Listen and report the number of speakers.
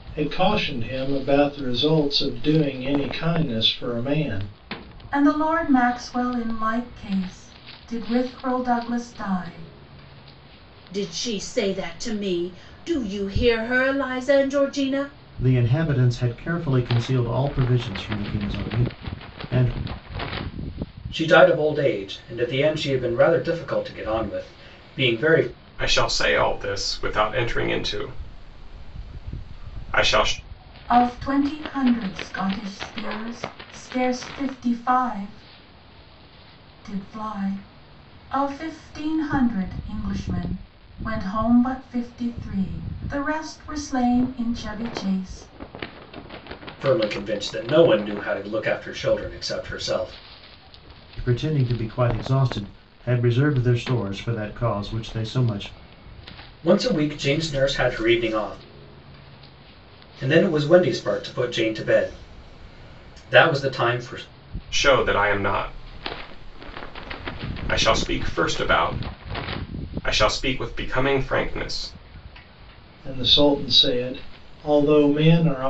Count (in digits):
6